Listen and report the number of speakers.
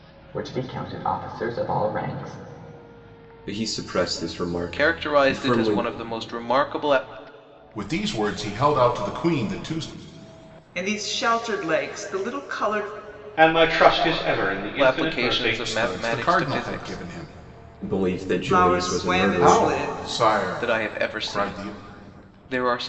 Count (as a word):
six